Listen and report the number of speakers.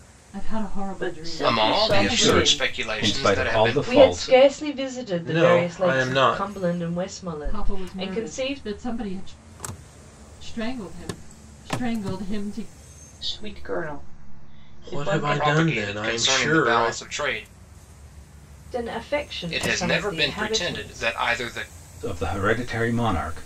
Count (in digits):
6